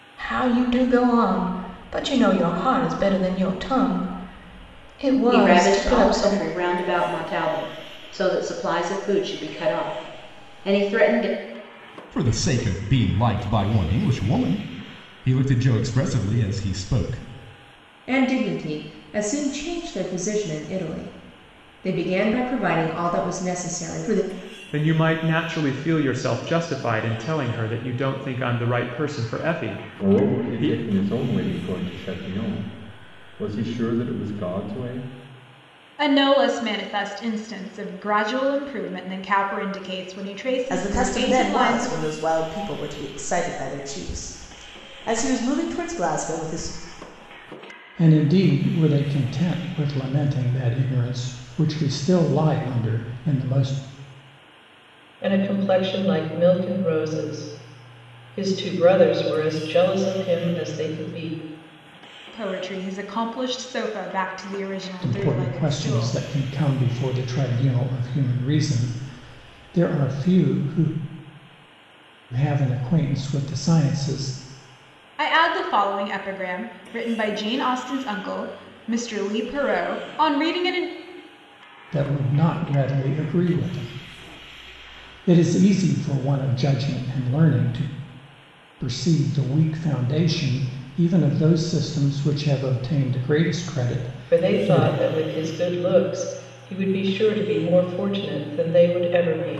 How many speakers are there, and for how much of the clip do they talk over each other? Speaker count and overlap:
10, about 5%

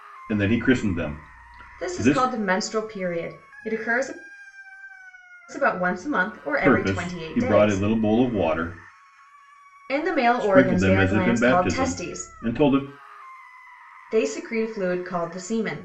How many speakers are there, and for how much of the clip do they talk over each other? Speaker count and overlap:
2, about 24%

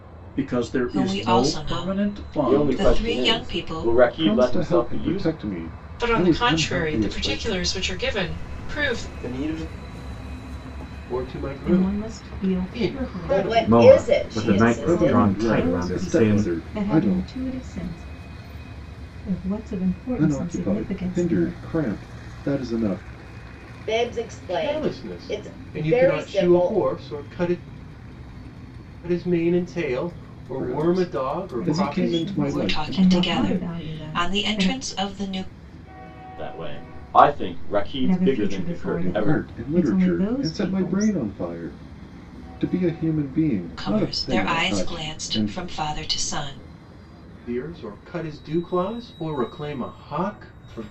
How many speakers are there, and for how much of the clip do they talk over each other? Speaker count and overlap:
10, about 51%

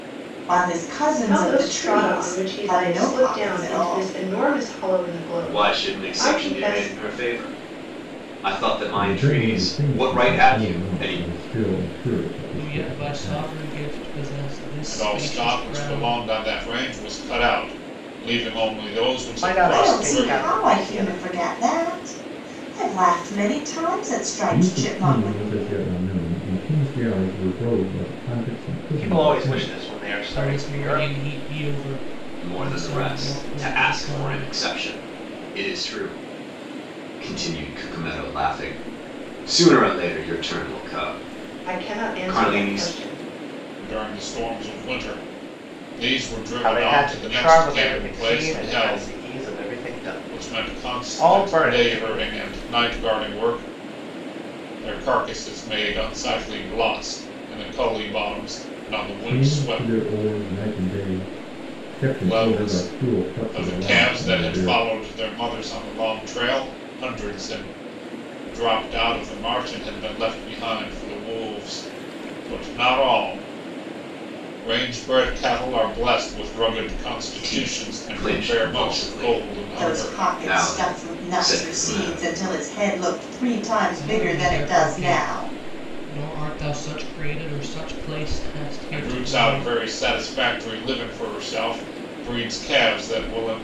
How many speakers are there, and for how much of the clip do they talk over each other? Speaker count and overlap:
7, about 35%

